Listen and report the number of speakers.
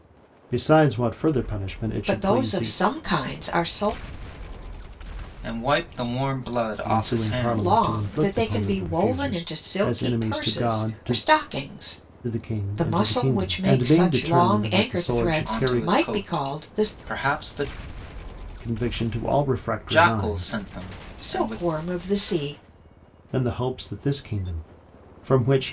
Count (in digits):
3